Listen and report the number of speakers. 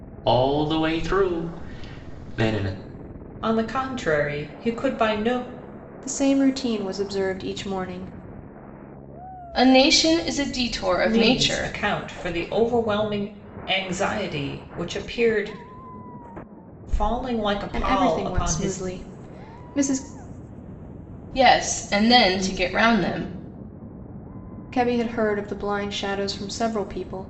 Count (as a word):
four